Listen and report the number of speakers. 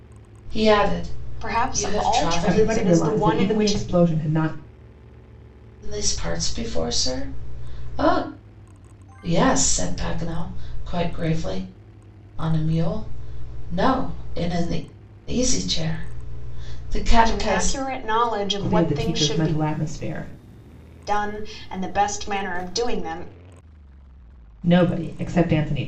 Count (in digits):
3